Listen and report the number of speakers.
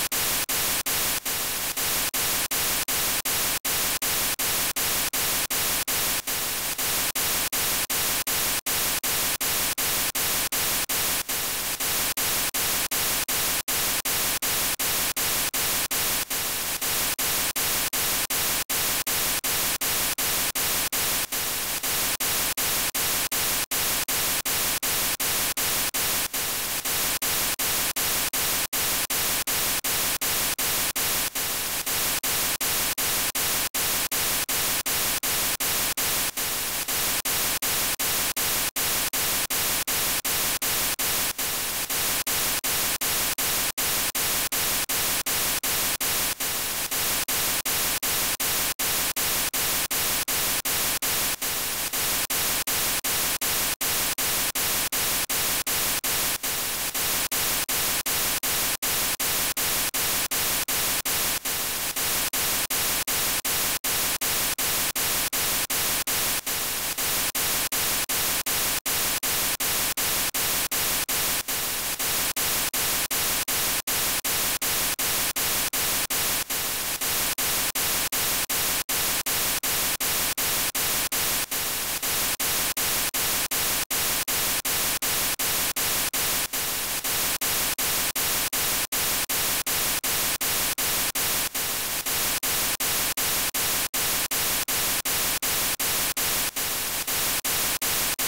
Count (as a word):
zero